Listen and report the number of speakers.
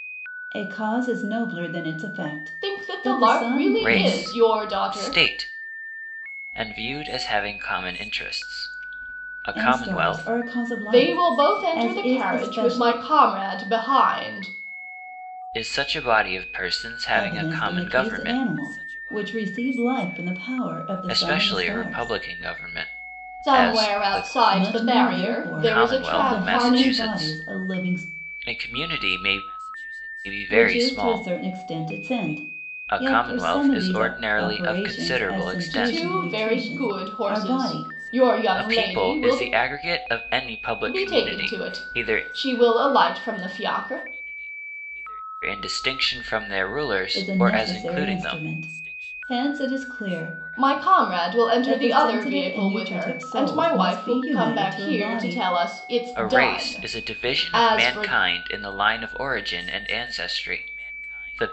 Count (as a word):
three